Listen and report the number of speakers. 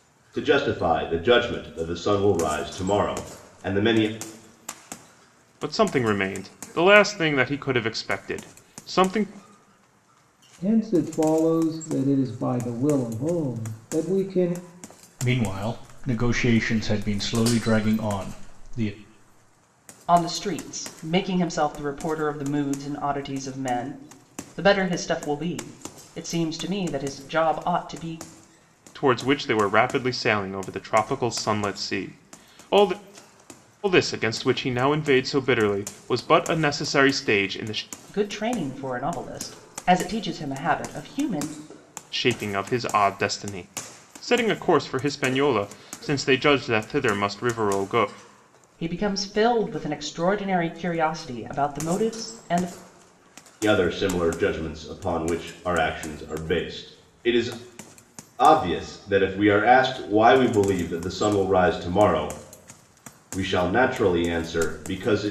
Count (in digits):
5